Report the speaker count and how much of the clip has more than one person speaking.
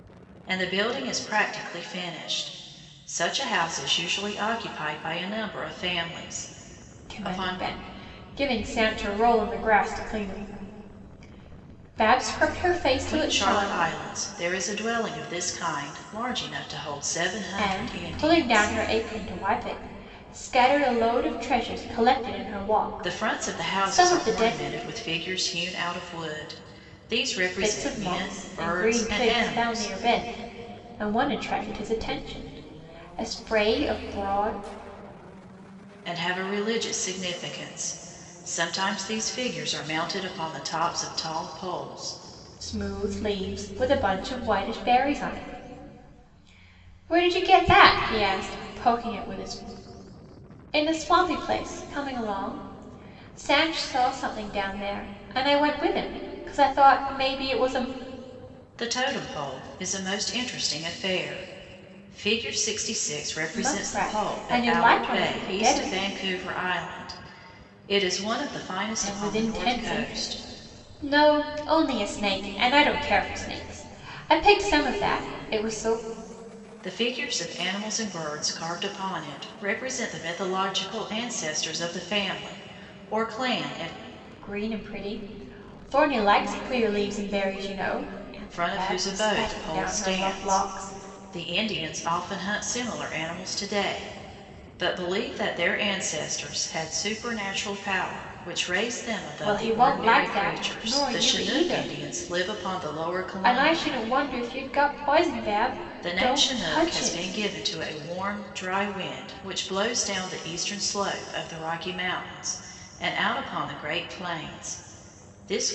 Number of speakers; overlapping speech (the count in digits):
2, about 15%